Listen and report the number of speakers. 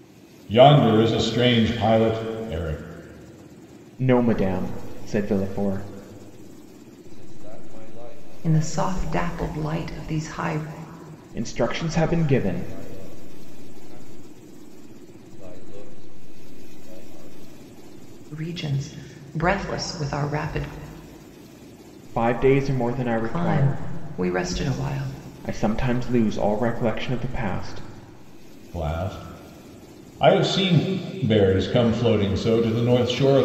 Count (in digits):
4